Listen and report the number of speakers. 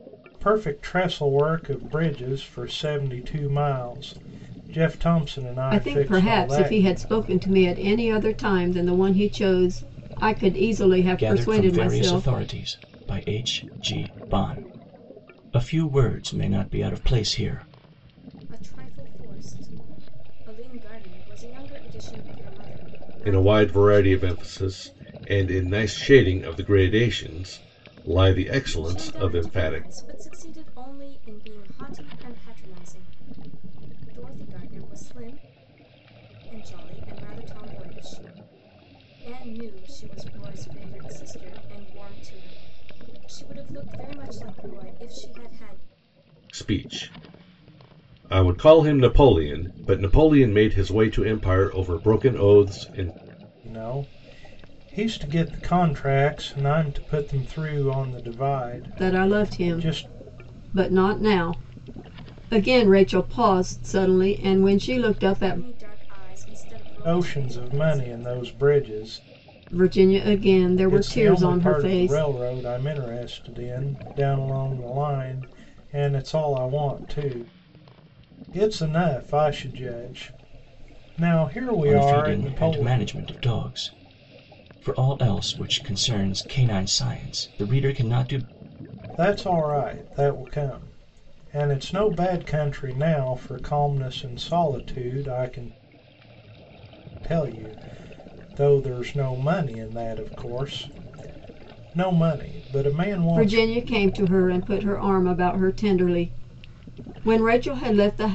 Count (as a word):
five